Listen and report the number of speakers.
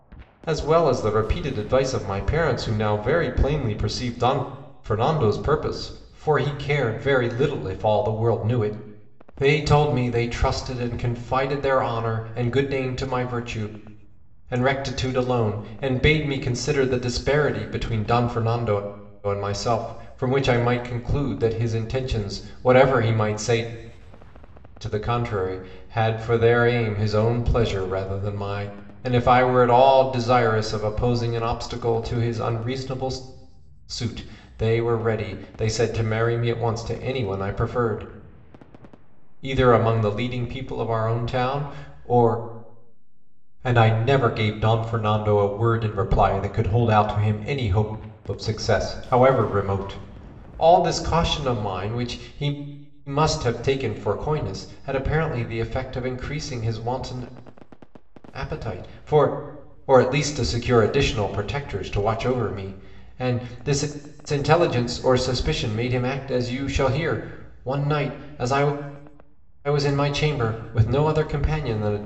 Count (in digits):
1